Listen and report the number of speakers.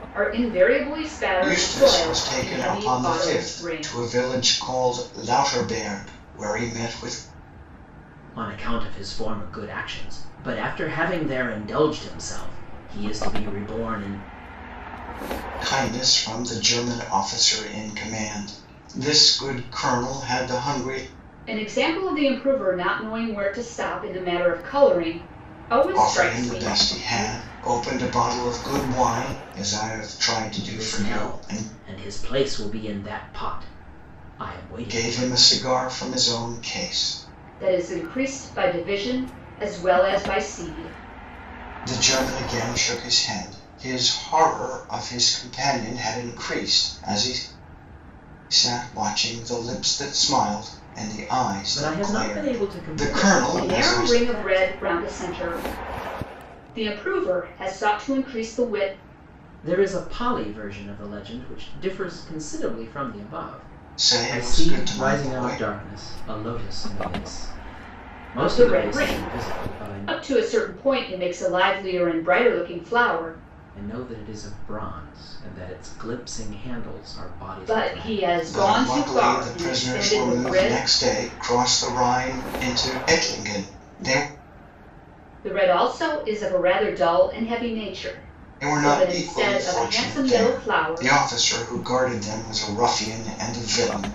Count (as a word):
three